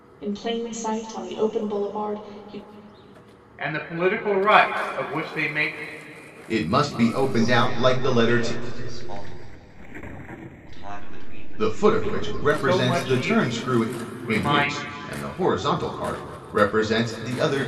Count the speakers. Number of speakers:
4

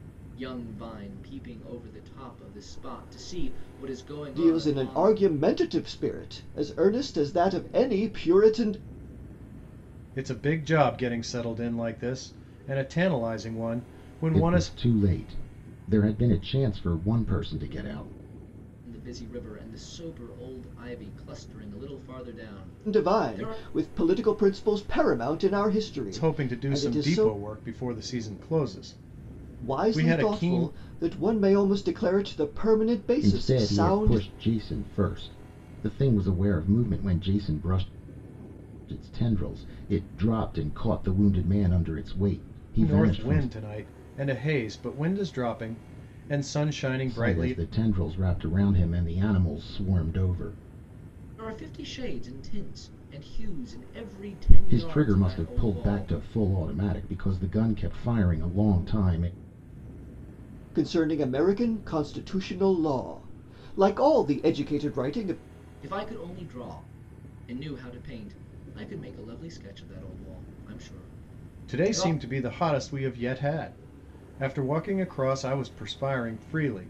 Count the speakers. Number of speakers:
4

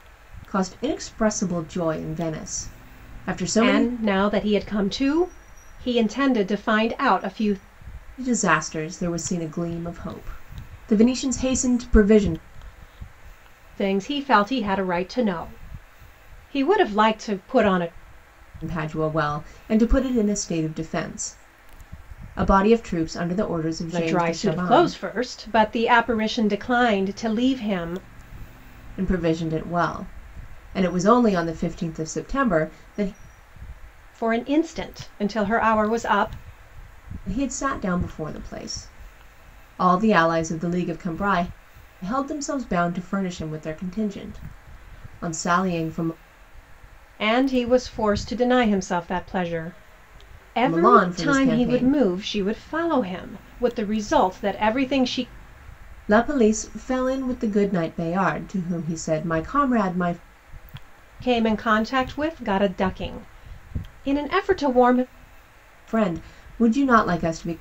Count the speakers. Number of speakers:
2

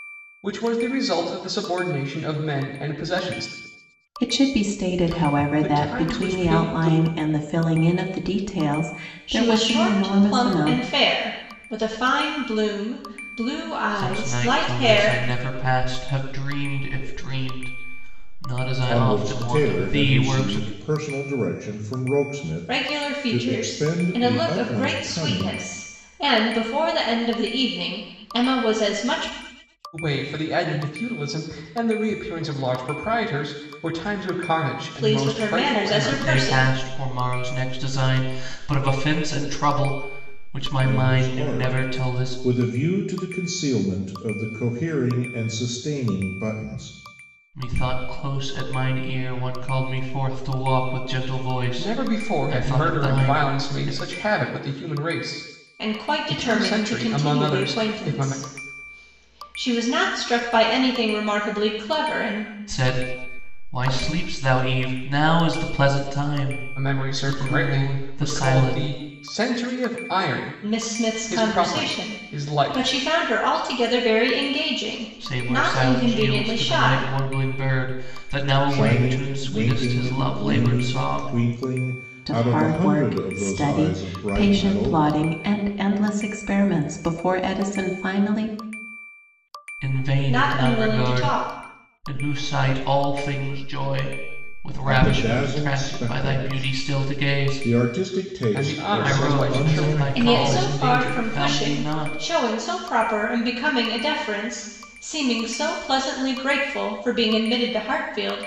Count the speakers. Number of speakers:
5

